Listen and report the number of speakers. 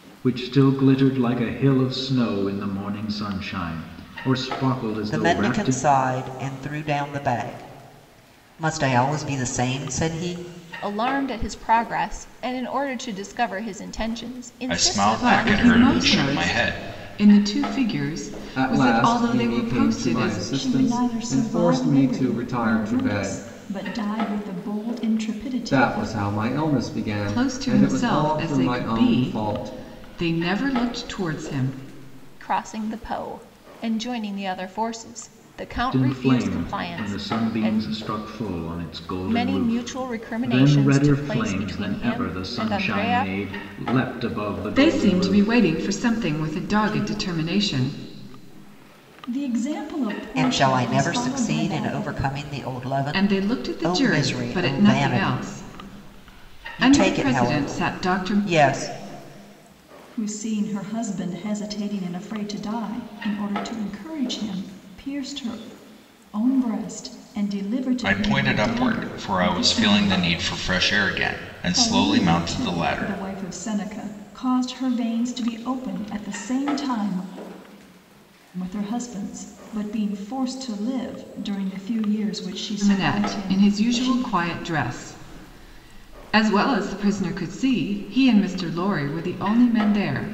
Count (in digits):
7